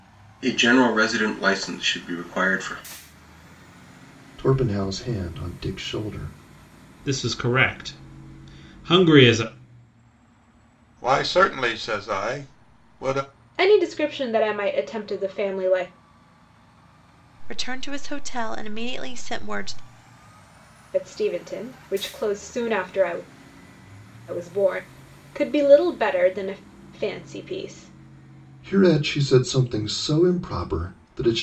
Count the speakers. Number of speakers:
6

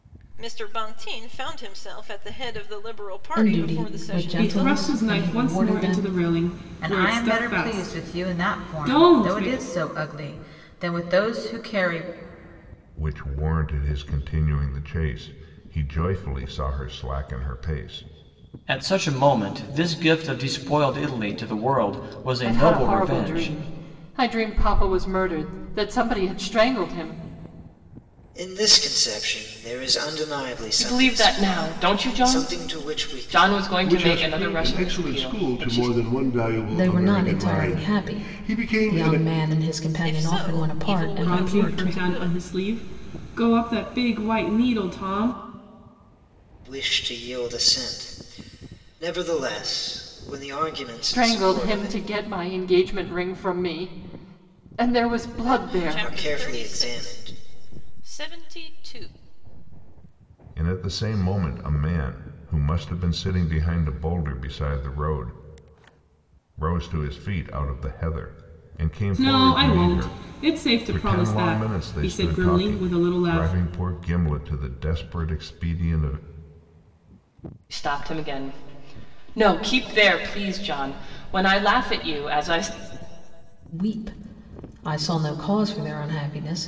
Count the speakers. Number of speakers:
10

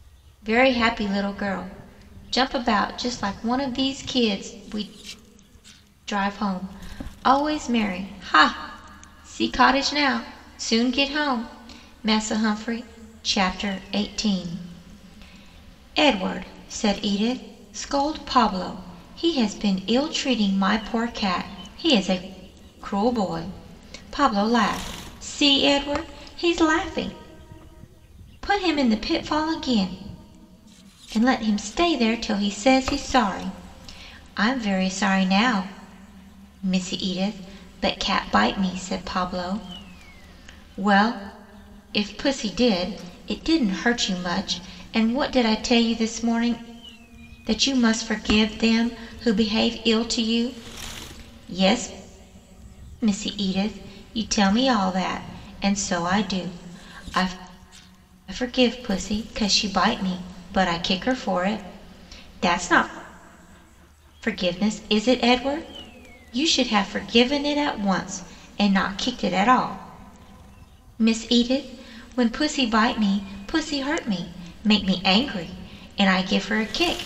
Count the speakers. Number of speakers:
1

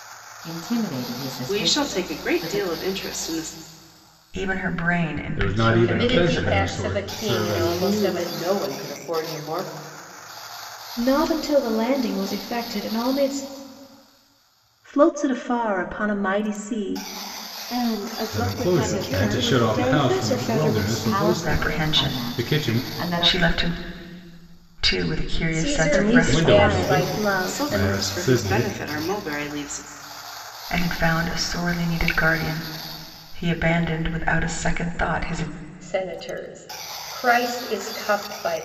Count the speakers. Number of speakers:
9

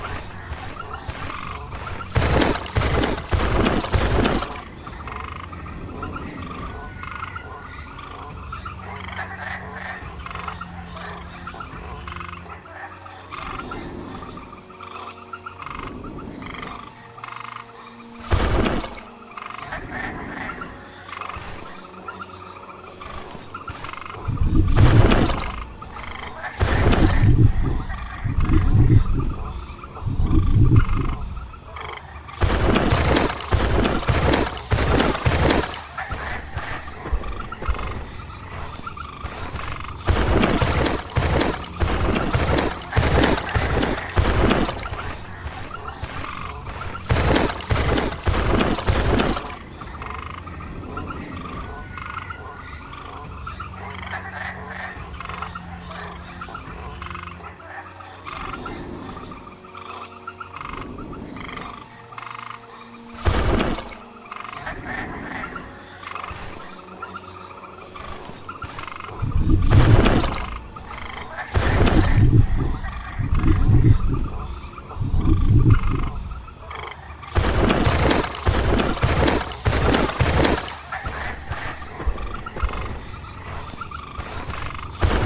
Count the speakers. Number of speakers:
0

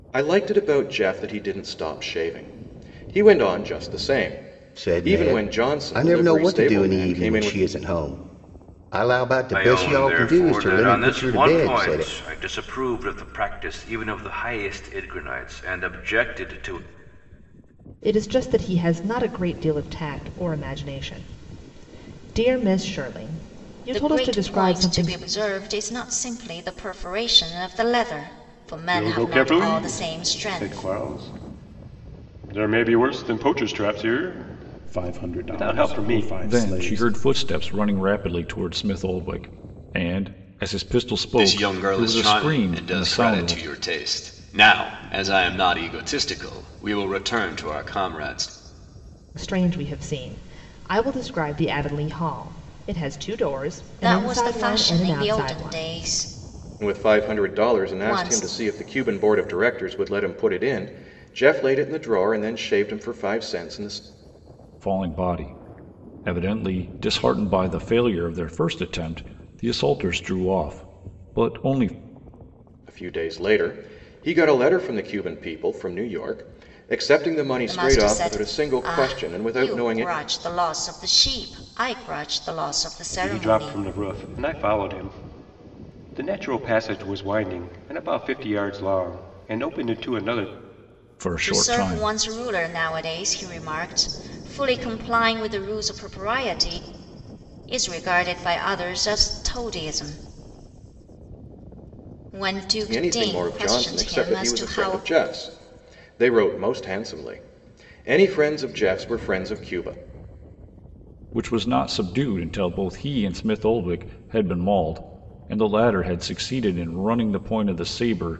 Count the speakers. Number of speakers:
9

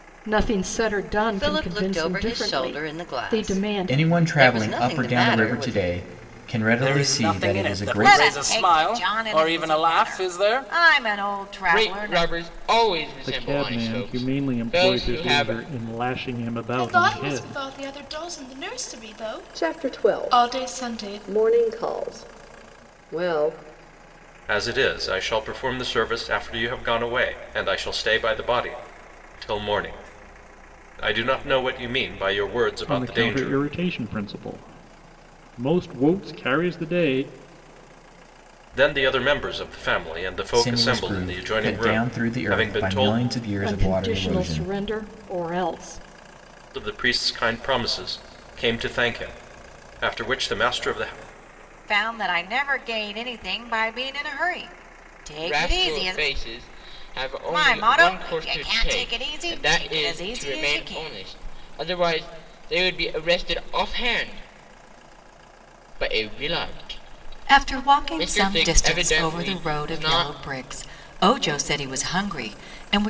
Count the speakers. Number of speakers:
10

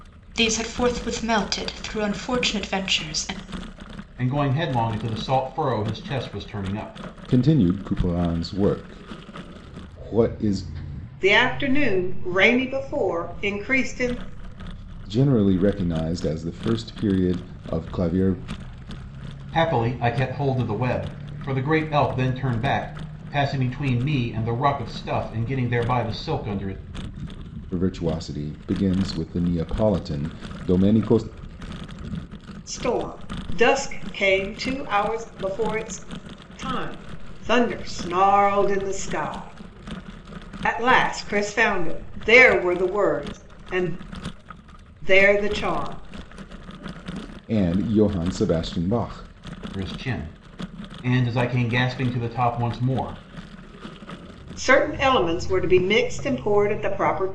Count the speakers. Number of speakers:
4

